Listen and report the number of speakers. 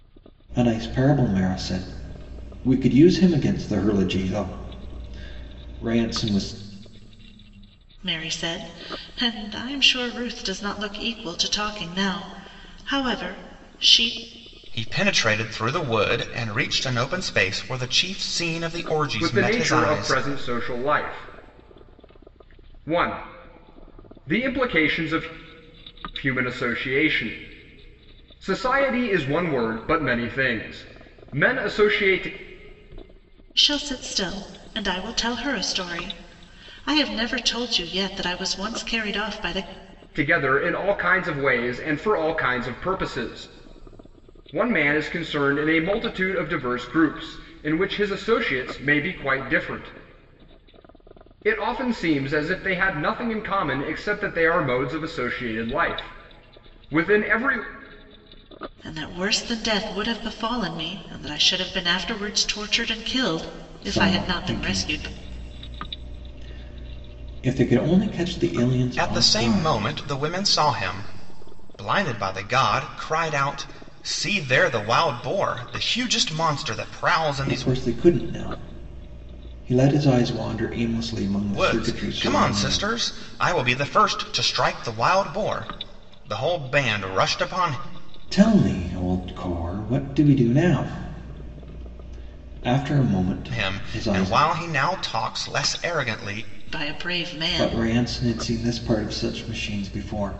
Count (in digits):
4